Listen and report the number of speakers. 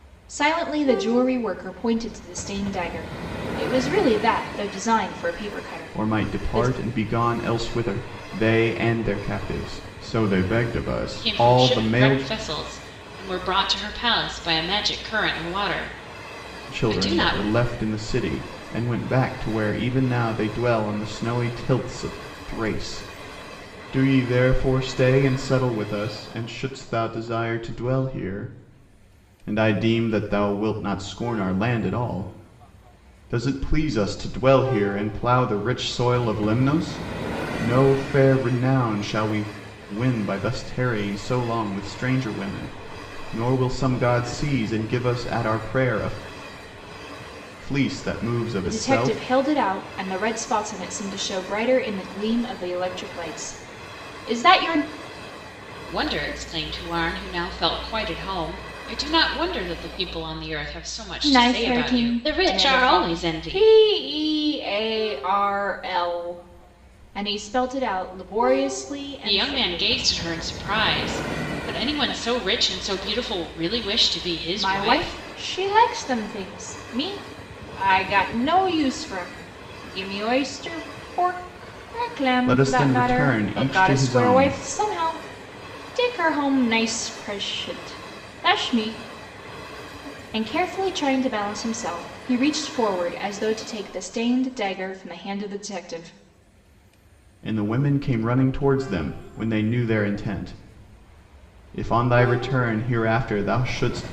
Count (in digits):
3